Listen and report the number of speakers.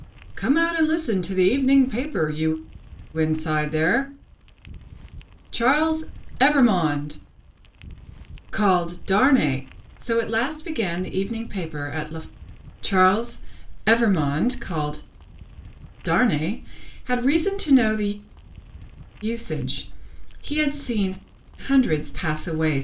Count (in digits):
1